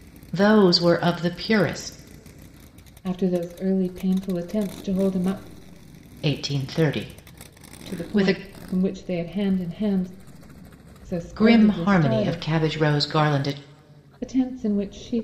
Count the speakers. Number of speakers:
two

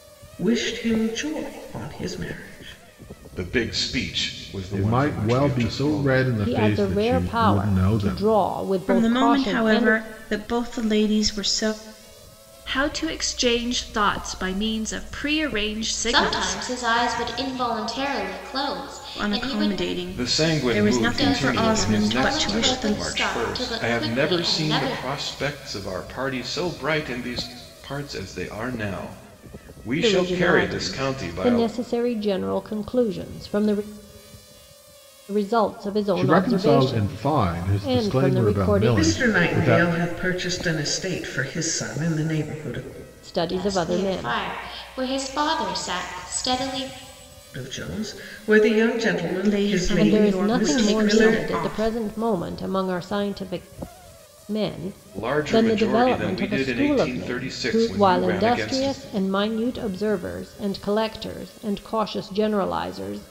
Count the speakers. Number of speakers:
seven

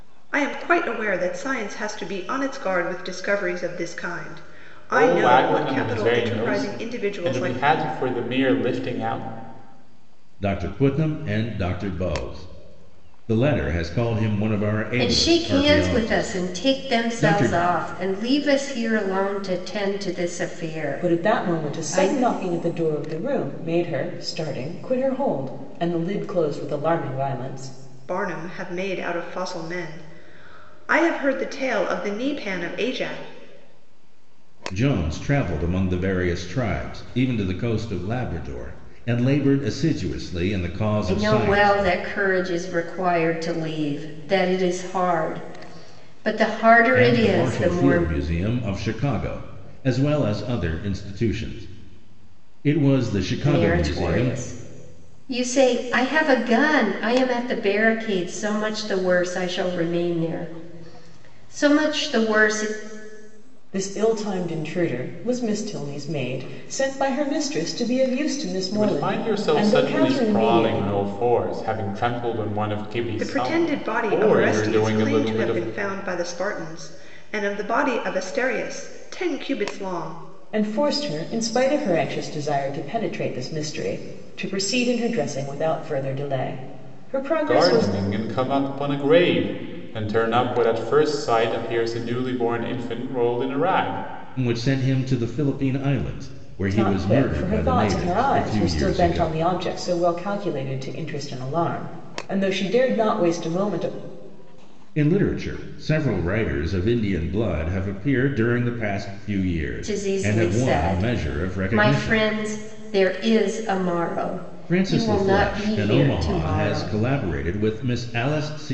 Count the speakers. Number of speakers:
five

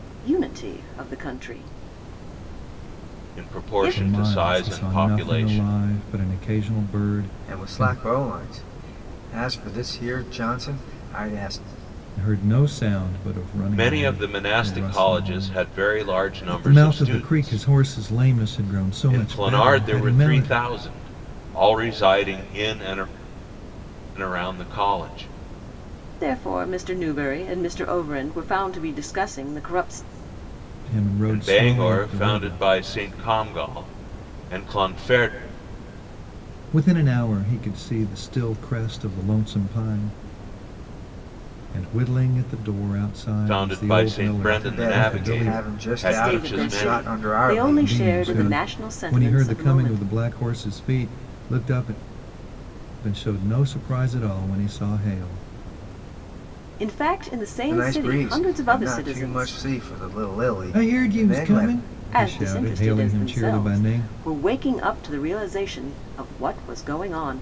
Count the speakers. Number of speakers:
four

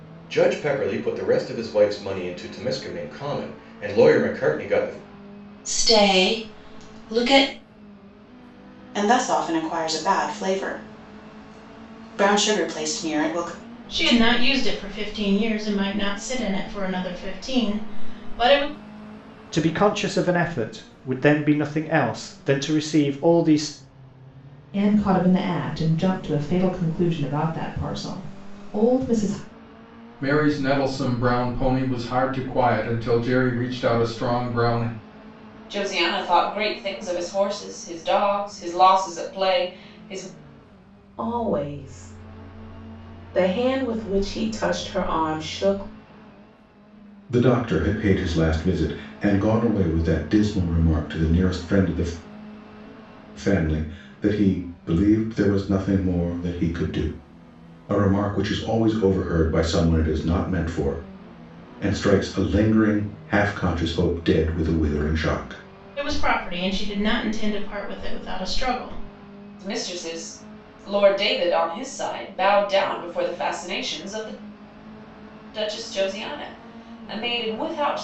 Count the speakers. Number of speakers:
ten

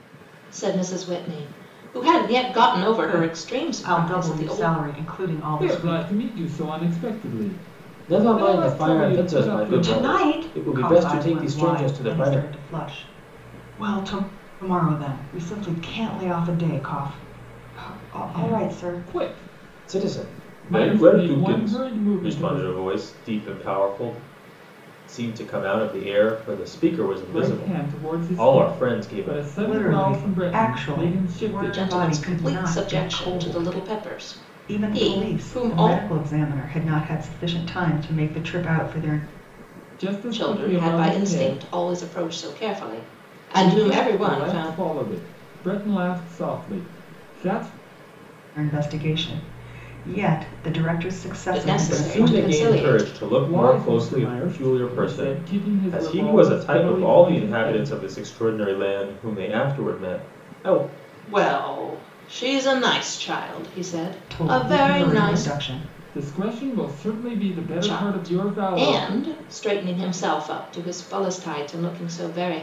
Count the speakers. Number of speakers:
four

